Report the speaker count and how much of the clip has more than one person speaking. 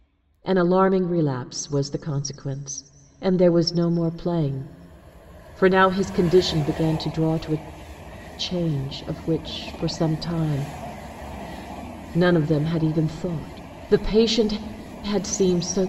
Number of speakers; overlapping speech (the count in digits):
1, no overlap